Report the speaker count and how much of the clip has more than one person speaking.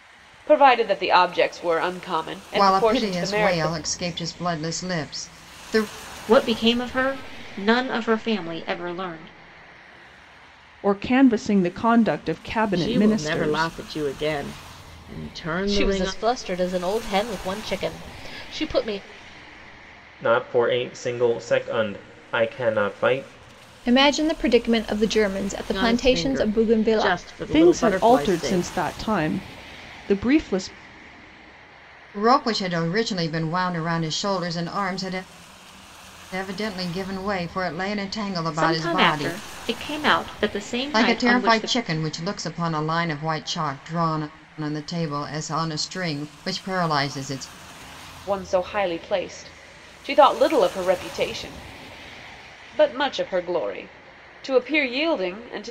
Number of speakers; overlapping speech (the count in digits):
8, about 13%